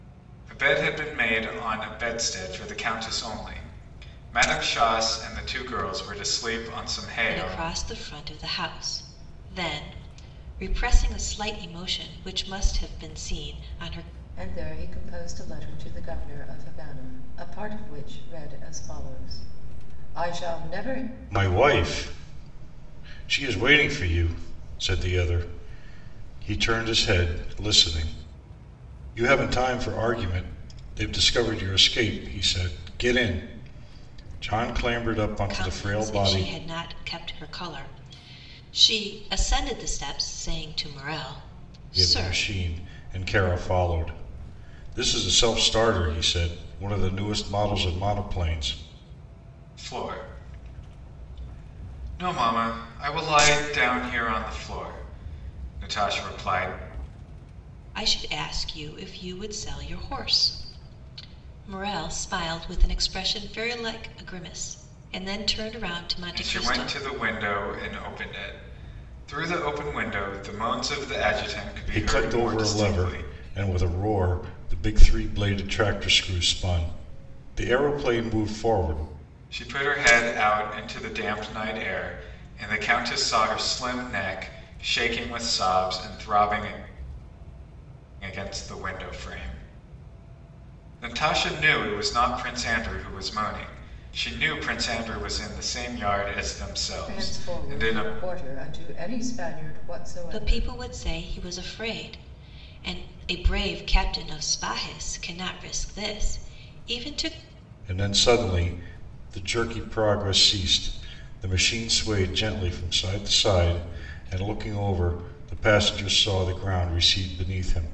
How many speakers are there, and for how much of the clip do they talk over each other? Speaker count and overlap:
4, about 5%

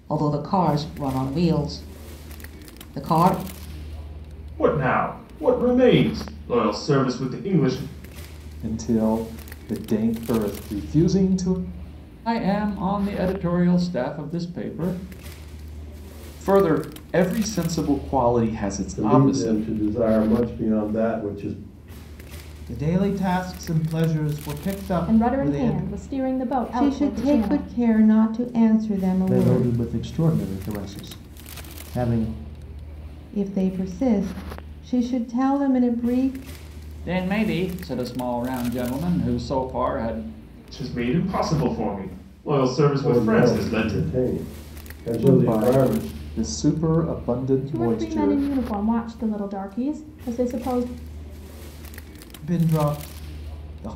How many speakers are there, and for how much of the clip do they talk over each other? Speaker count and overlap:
10, about 11%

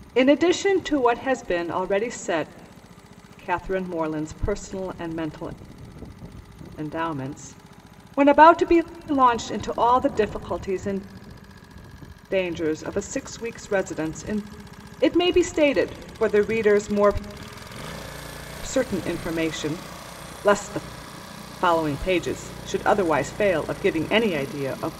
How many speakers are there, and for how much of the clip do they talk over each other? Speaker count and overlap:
1, no overlap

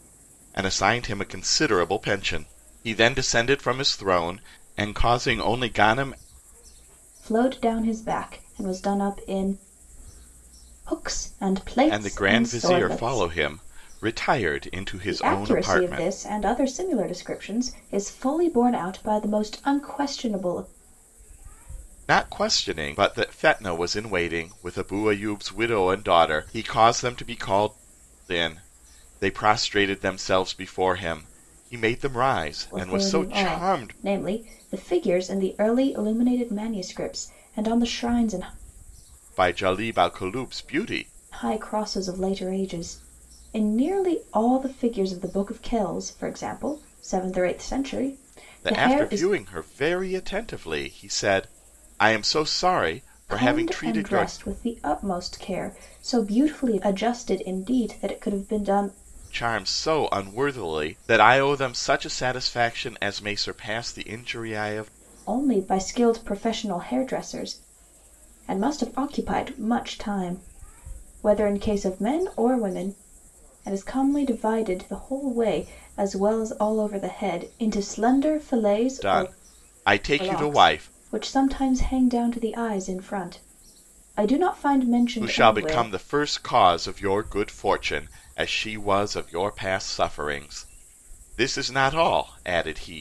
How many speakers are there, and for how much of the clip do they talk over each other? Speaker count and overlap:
2, about 8%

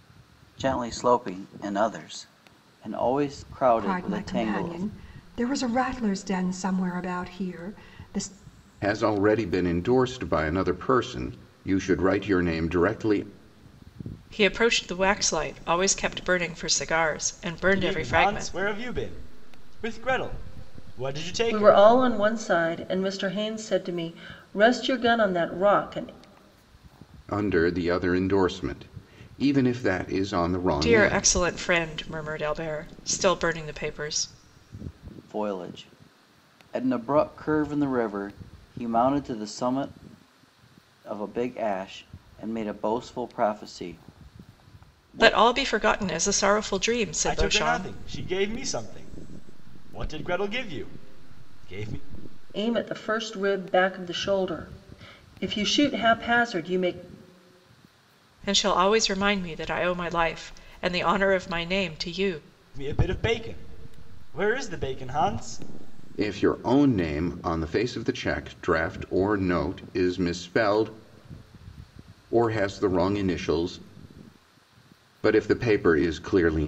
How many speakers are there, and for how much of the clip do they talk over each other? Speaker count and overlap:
6, about 5%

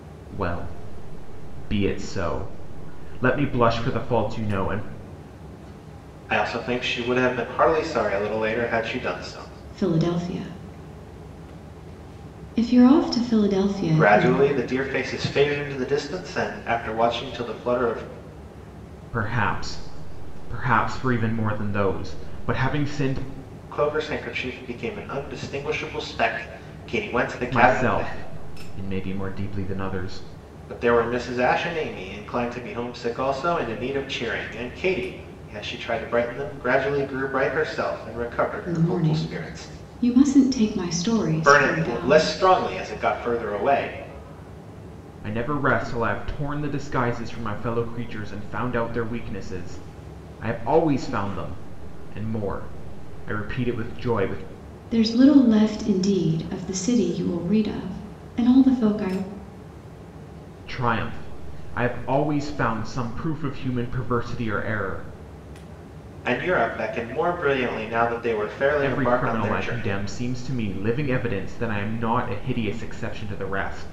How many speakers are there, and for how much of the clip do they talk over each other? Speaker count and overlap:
3, about 6%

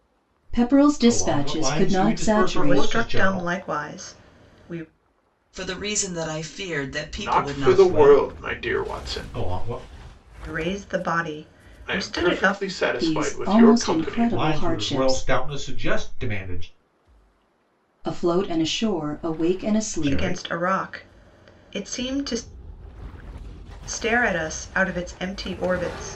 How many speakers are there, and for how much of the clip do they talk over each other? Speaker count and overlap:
5, about 32%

